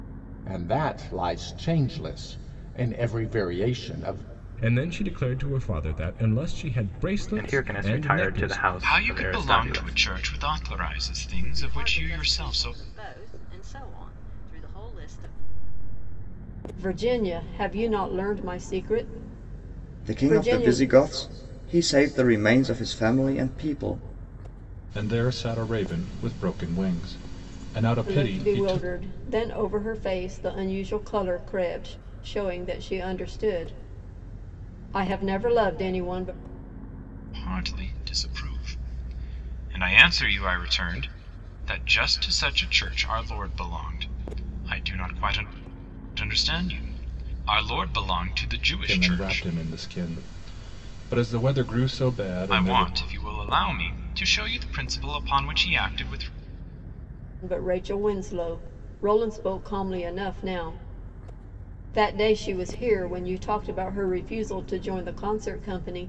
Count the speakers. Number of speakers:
eight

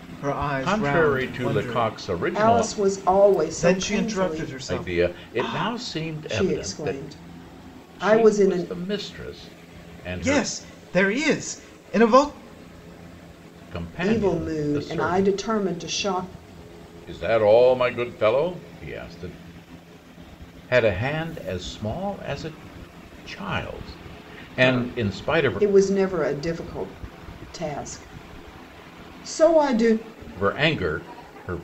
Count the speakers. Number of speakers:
three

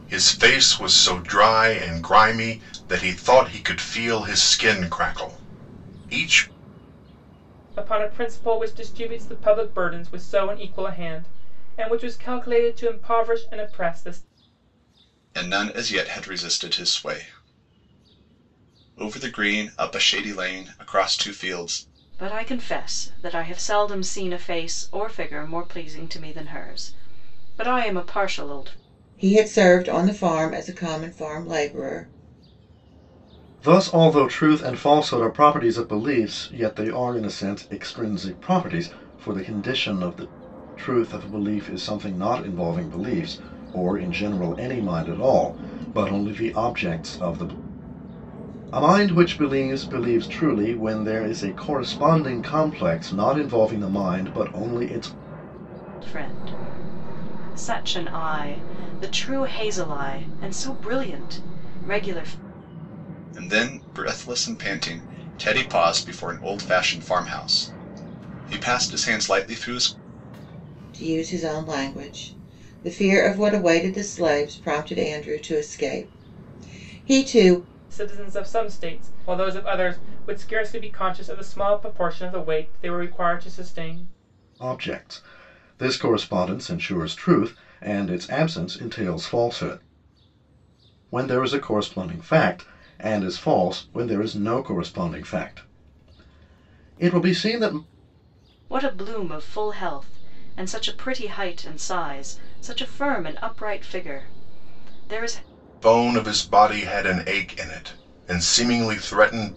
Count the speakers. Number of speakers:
six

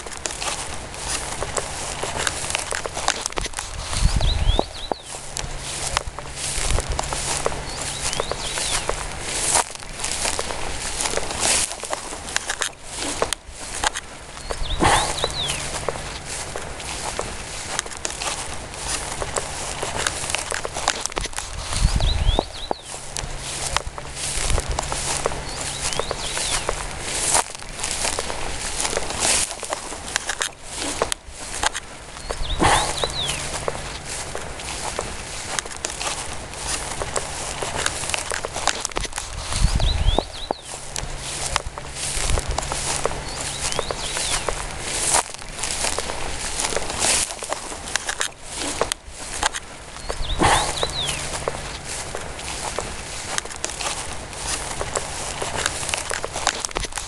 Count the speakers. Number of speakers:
zero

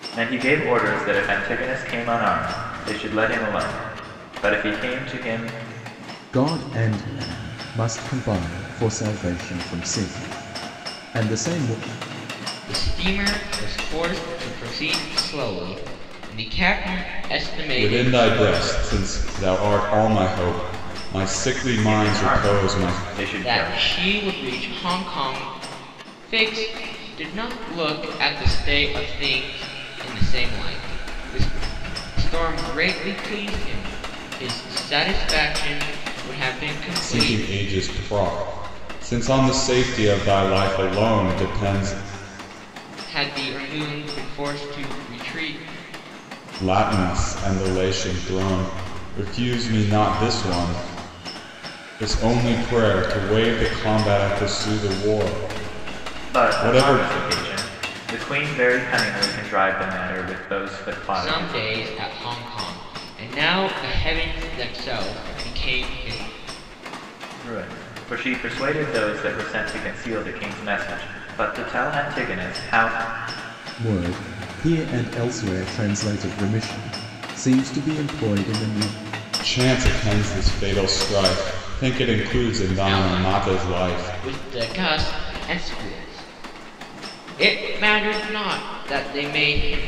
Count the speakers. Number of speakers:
four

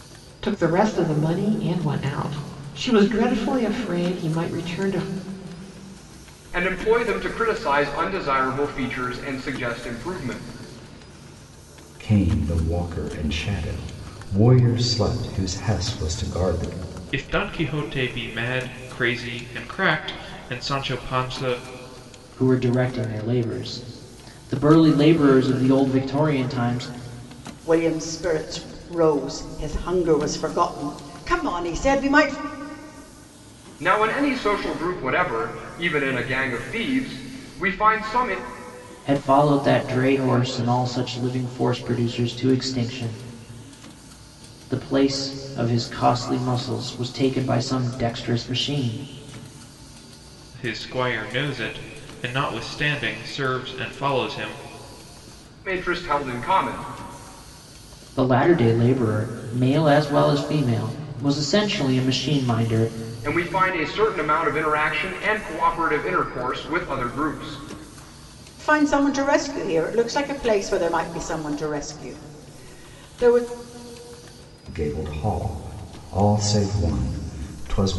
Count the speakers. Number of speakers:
six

